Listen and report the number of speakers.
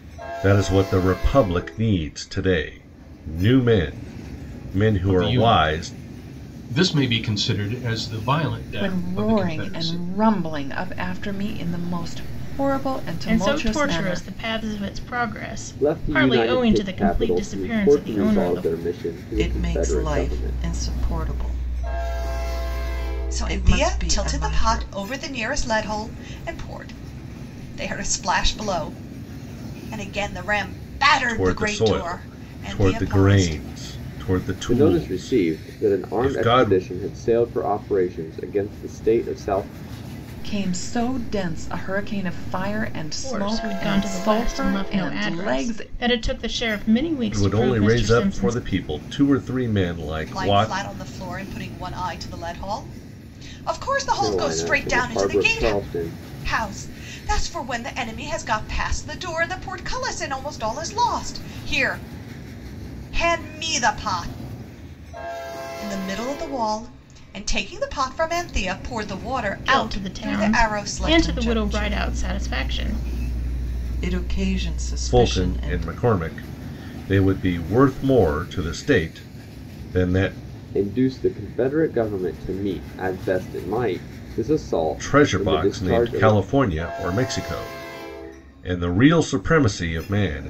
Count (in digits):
7